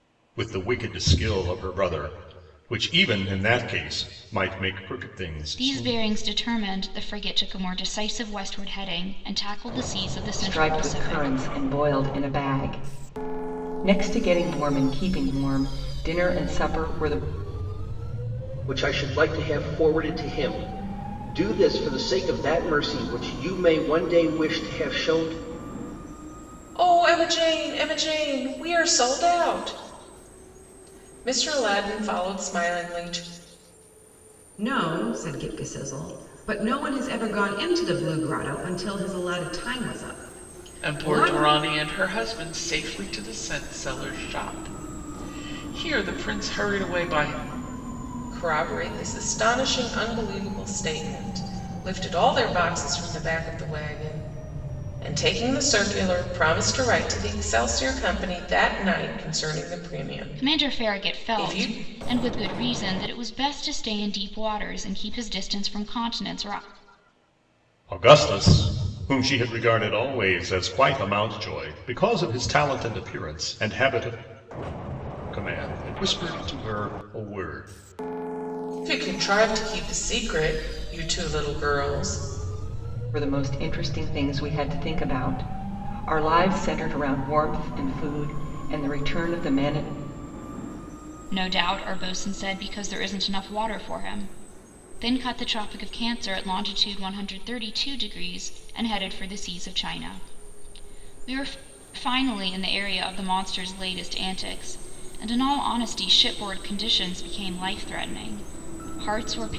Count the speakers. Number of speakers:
7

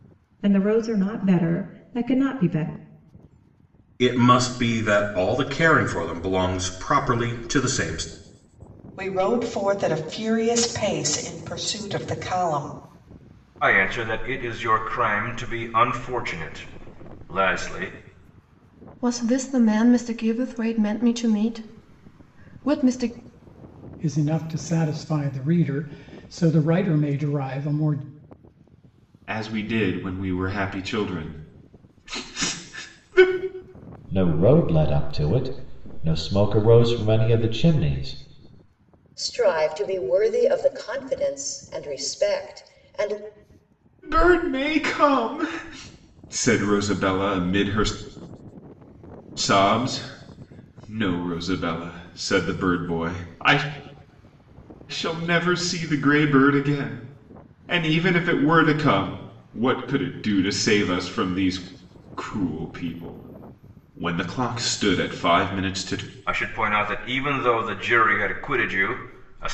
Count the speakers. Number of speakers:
9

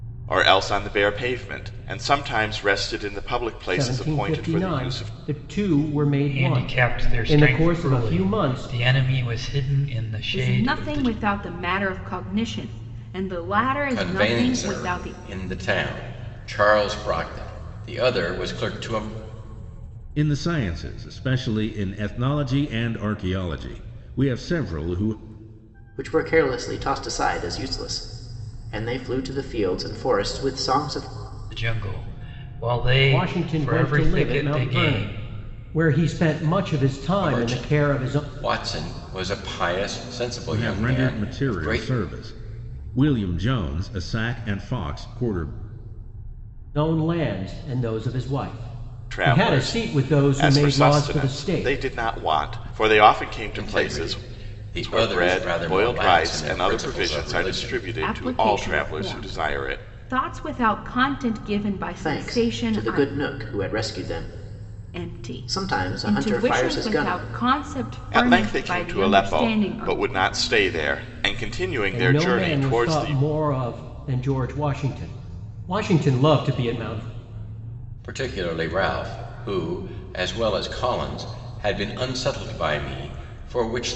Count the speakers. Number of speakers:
7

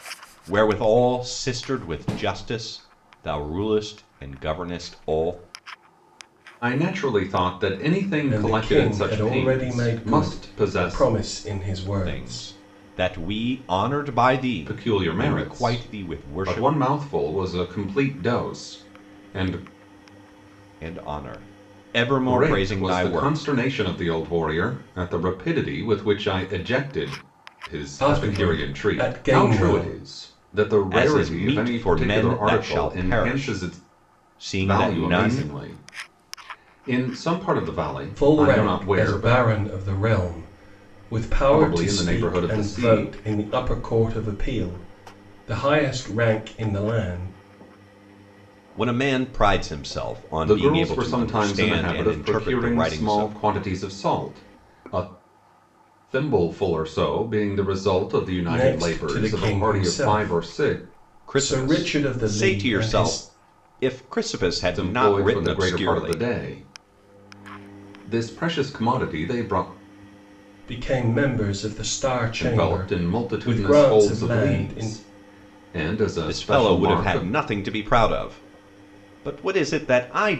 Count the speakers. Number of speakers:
3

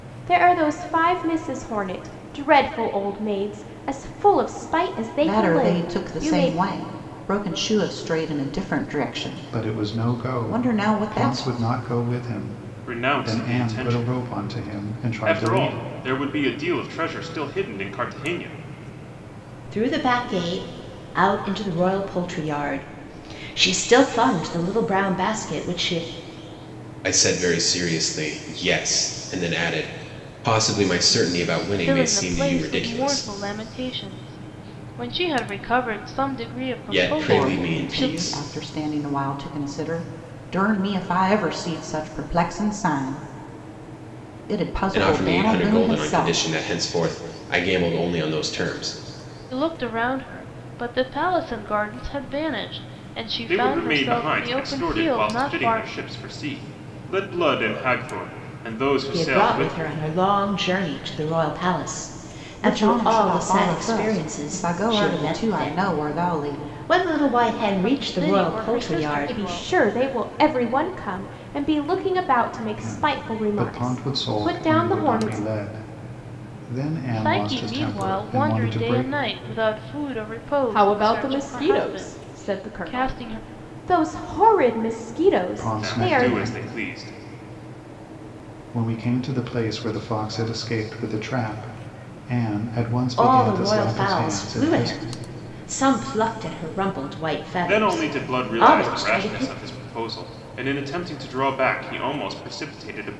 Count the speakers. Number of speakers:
7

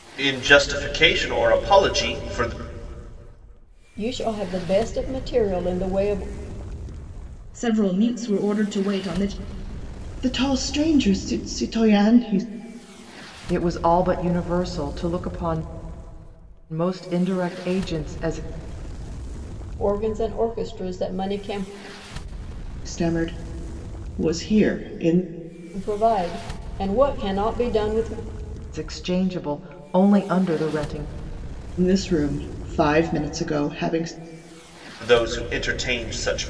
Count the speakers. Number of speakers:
5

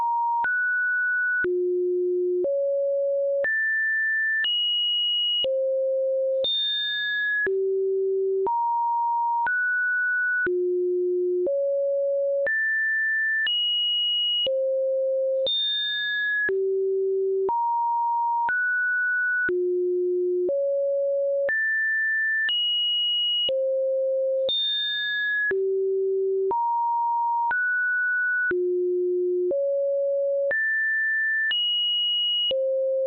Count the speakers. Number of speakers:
0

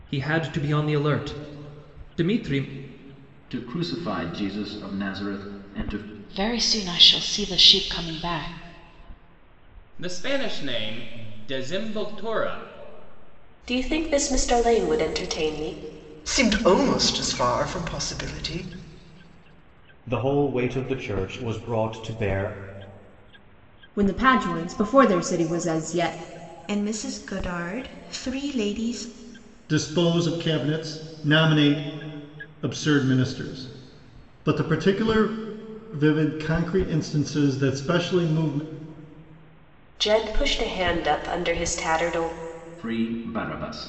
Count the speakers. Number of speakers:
10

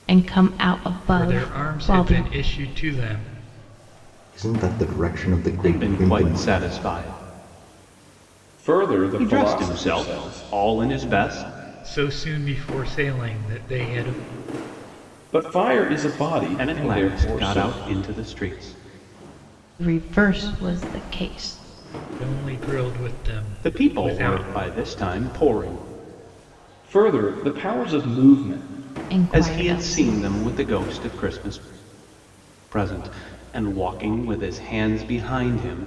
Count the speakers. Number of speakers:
5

